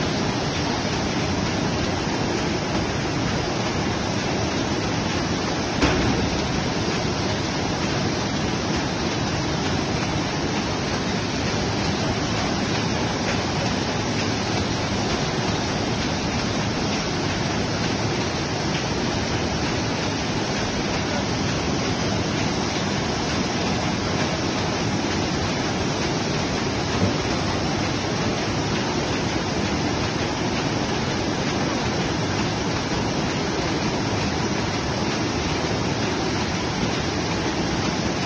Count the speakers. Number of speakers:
0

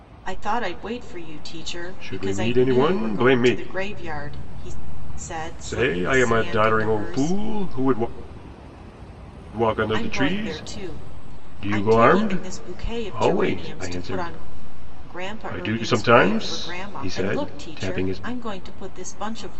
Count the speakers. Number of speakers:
2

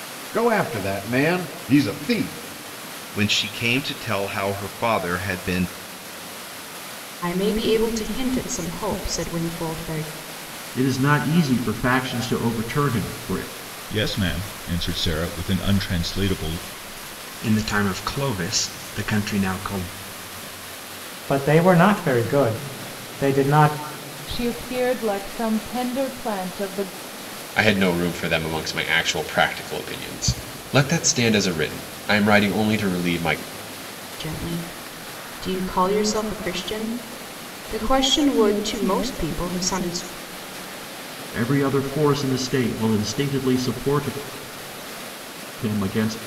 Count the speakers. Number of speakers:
9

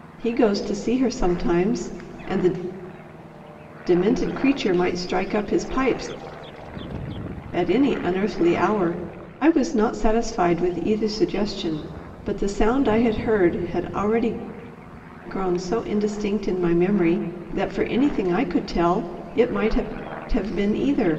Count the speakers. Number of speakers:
1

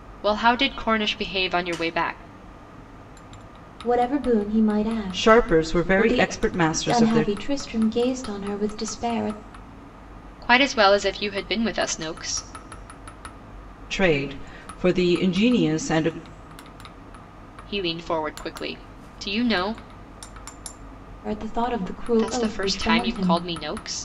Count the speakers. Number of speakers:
3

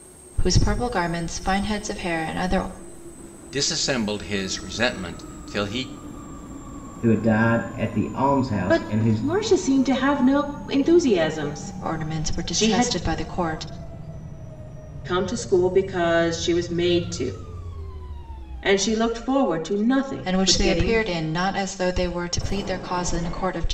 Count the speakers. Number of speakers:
4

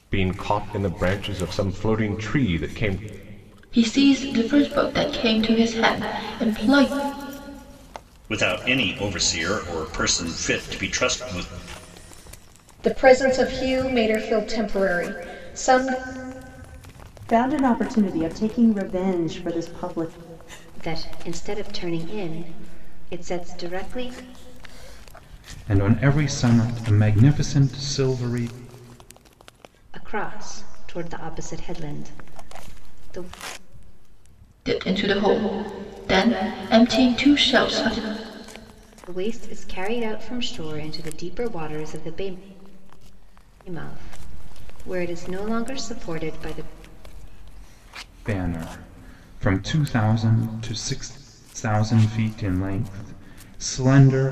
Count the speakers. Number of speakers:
7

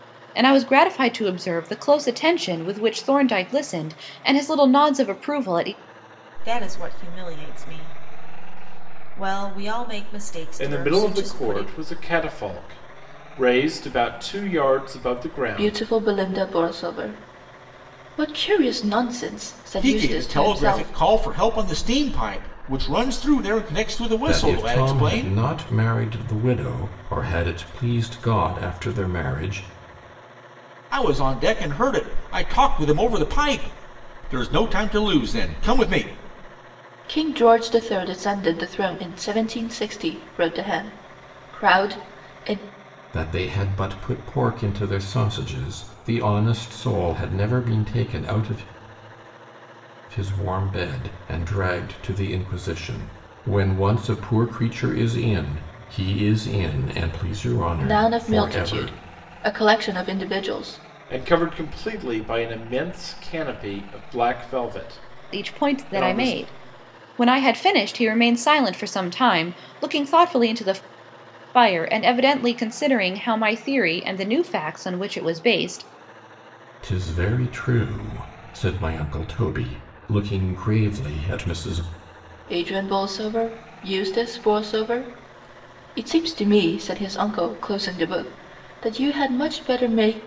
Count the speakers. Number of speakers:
6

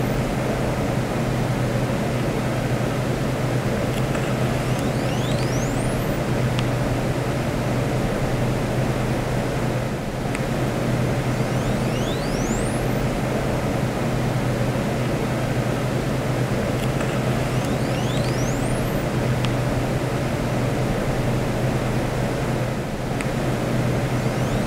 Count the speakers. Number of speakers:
0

